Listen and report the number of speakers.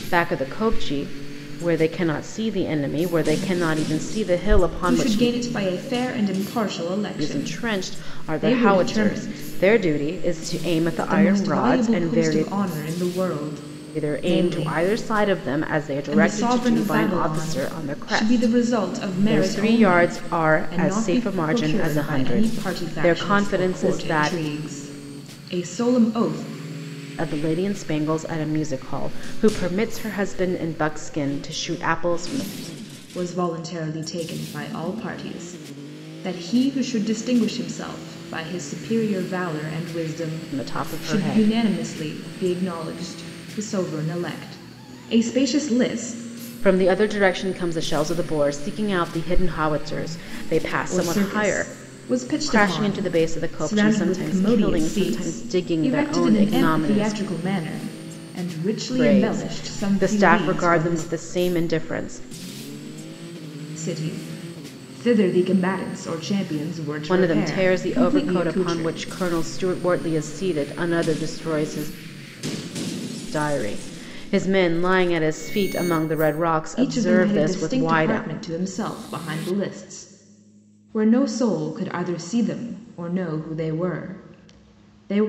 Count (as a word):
two